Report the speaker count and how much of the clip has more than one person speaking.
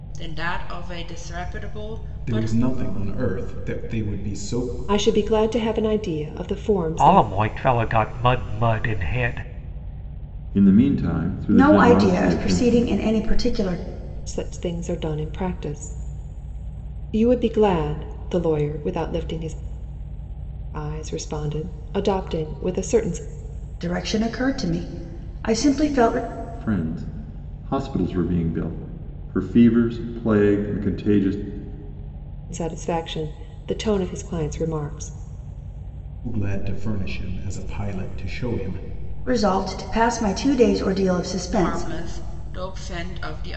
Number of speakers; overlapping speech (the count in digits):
6, about 6%